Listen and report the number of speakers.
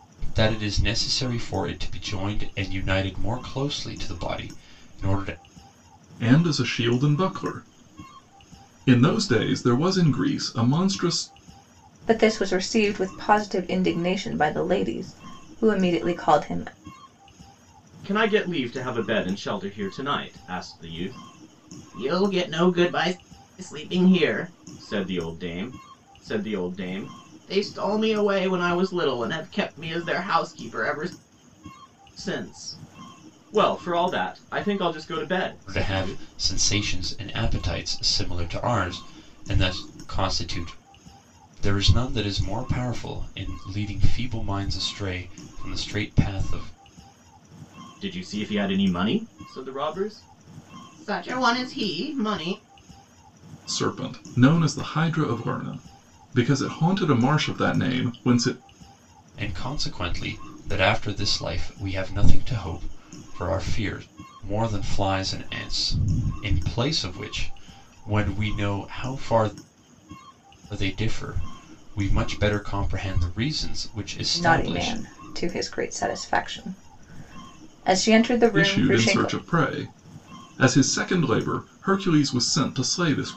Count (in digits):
4